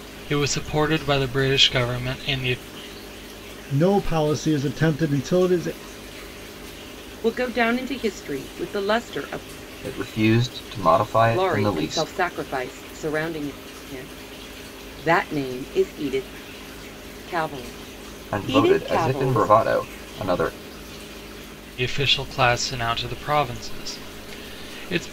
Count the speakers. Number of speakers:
4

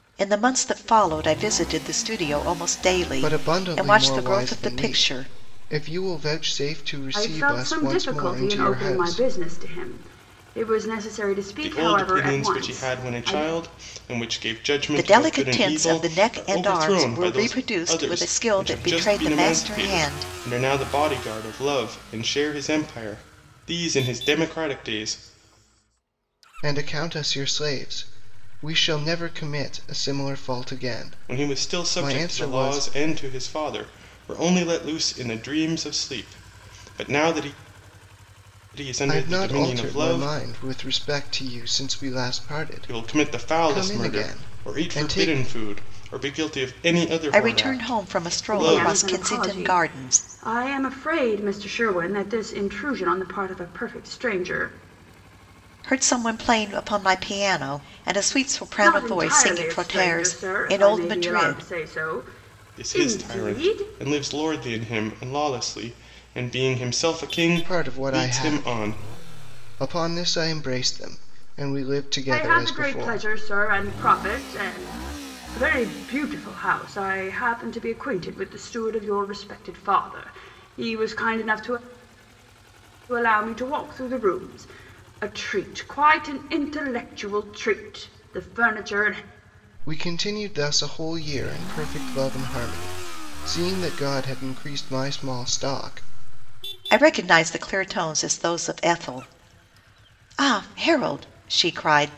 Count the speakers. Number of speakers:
4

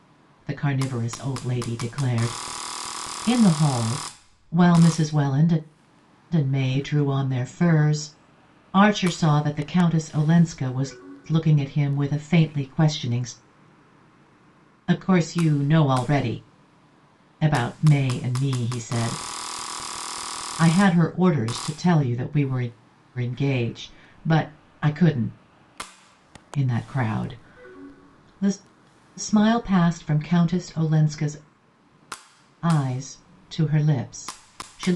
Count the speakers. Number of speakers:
1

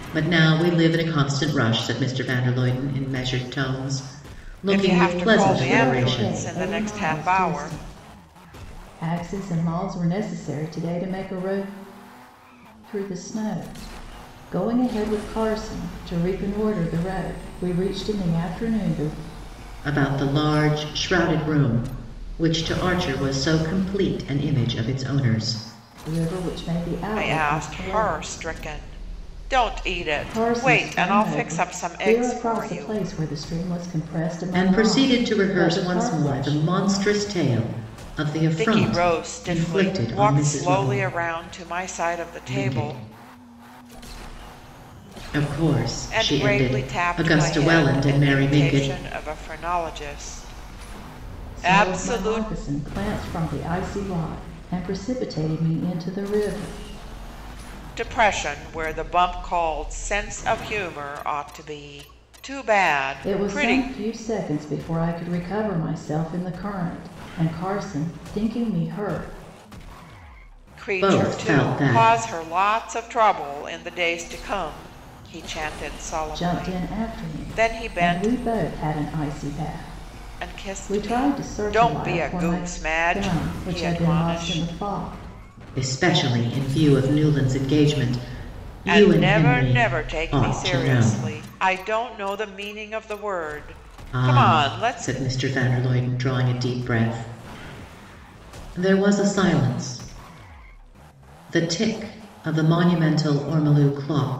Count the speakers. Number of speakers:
3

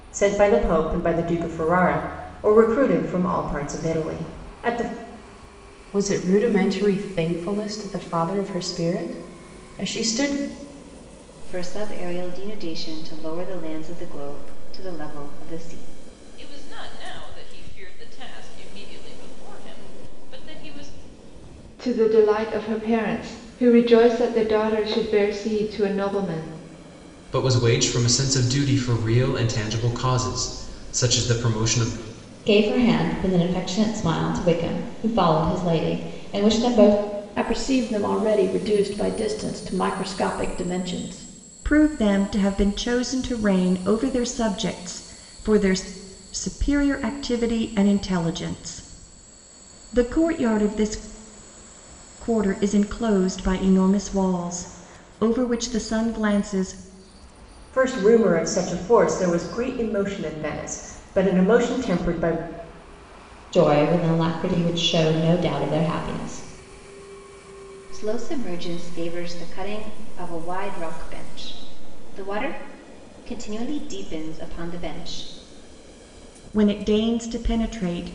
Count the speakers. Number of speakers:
9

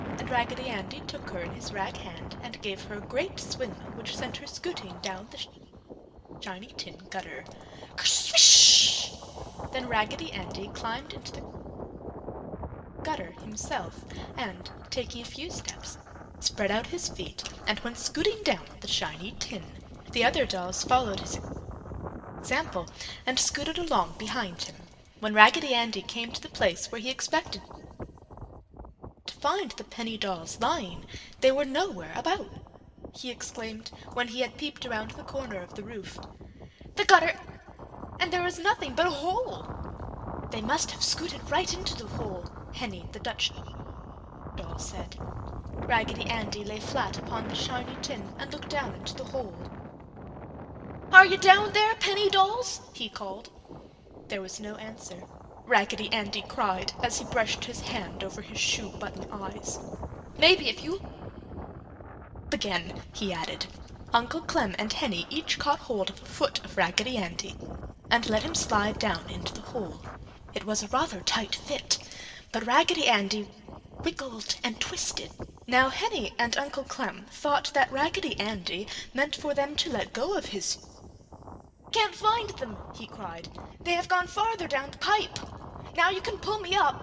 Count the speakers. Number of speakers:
1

